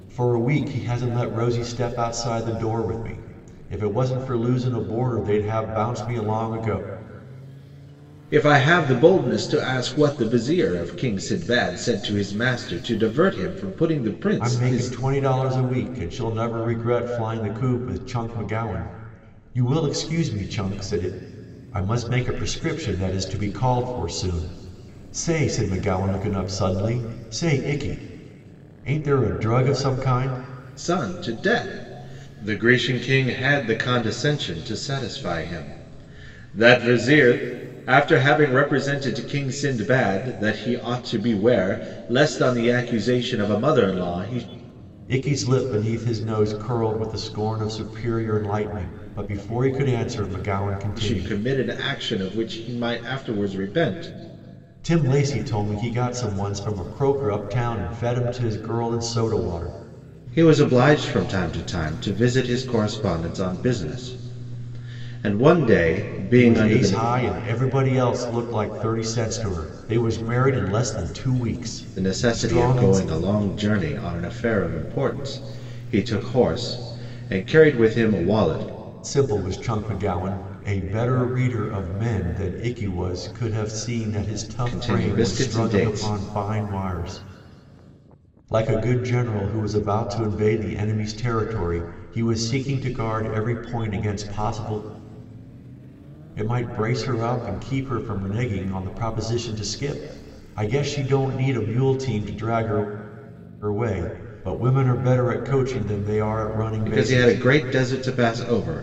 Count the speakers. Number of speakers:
2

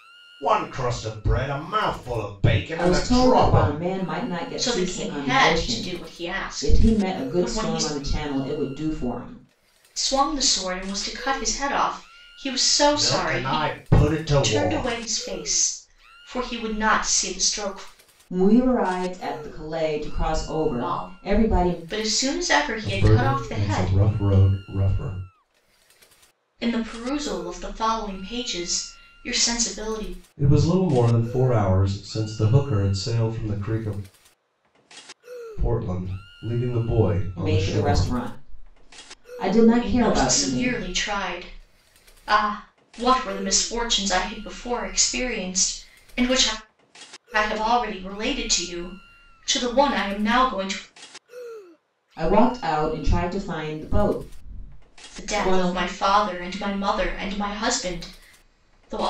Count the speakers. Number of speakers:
3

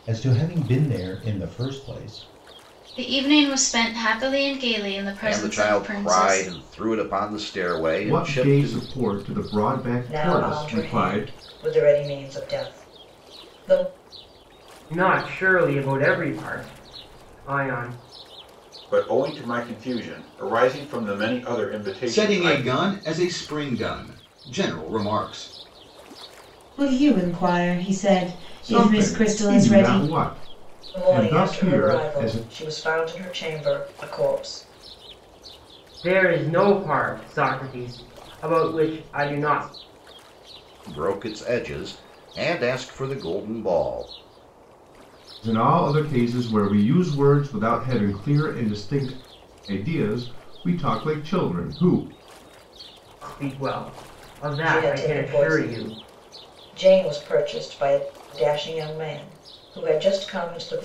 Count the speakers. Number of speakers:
9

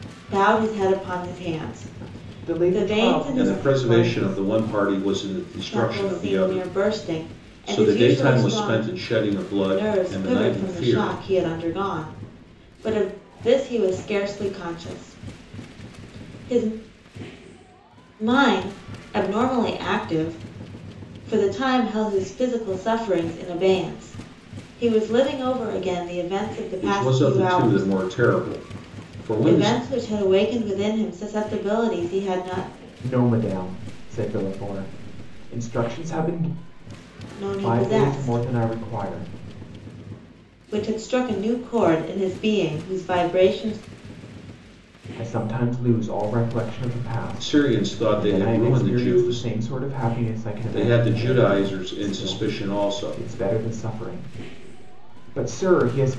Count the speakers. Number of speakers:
3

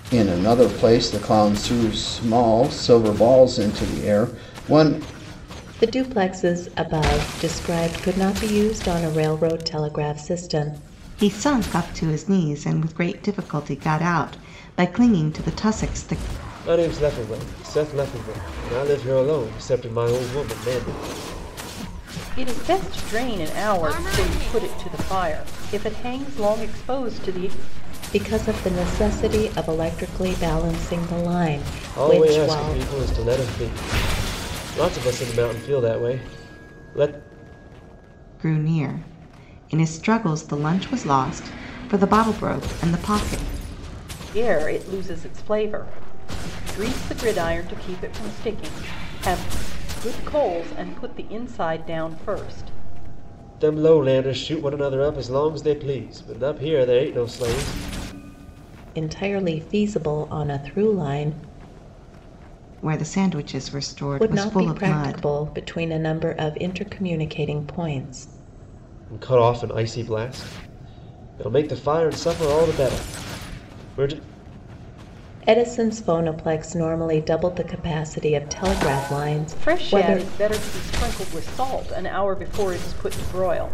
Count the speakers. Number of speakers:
5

